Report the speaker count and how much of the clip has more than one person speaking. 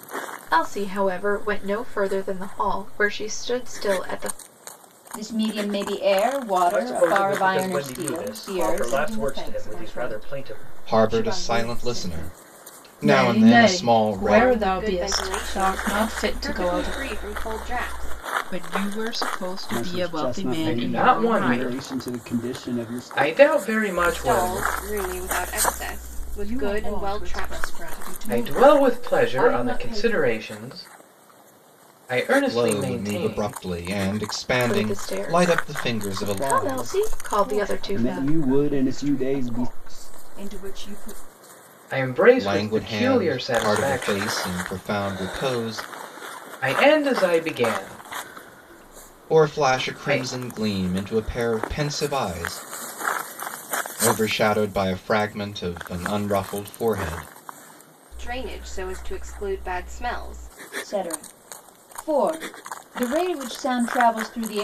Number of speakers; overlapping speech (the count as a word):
ten, about 40%